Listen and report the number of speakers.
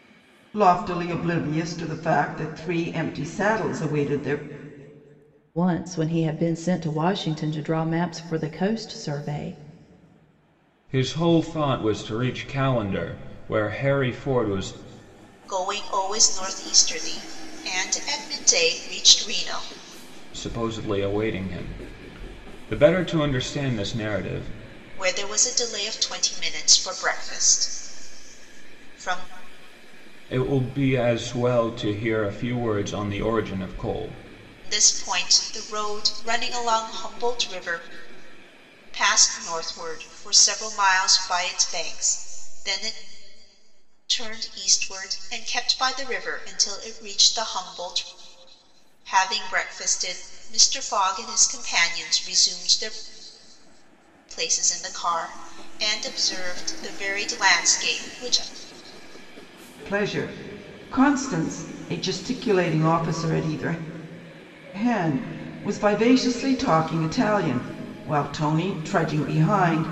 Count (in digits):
4